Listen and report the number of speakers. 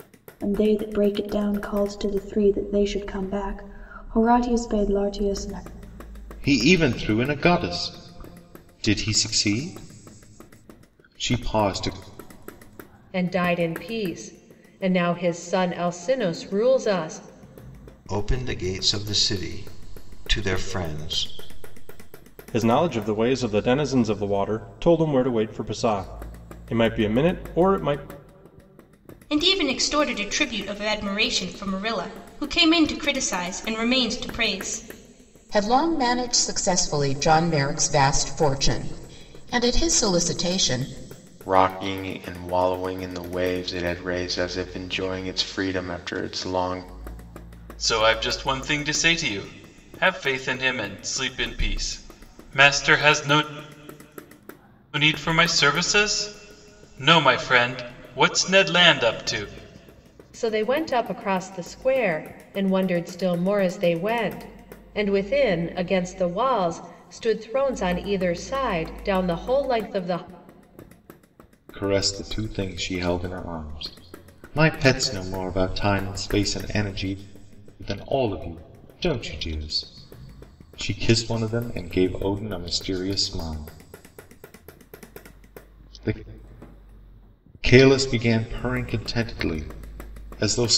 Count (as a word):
nine